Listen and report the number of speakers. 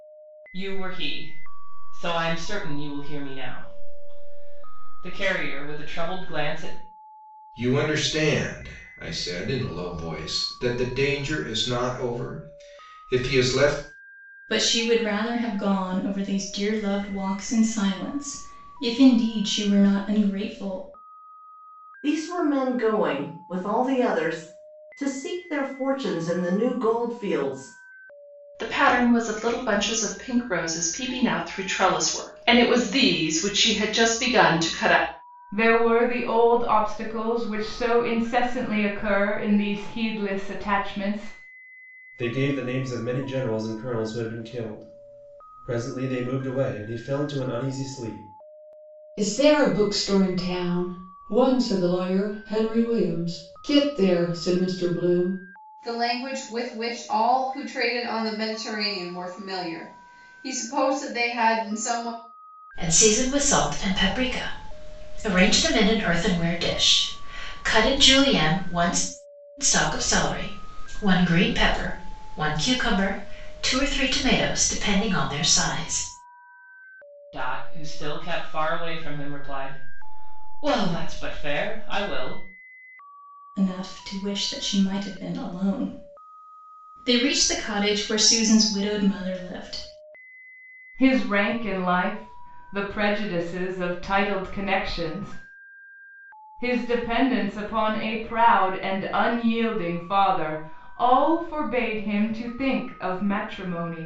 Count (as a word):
ten